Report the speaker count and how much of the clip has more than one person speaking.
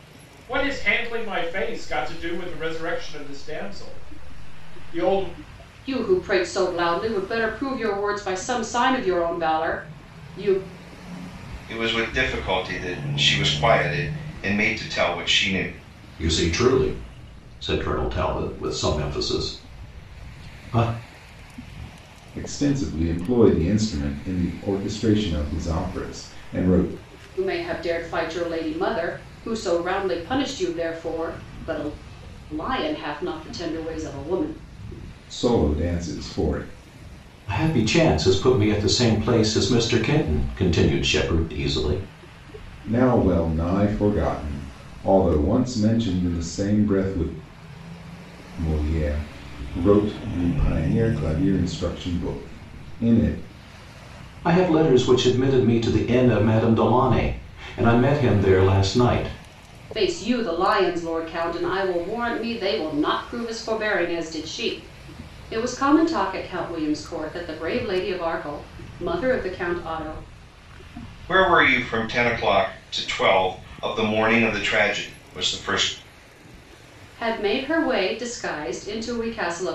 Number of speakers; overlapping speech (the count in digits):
5, no overlap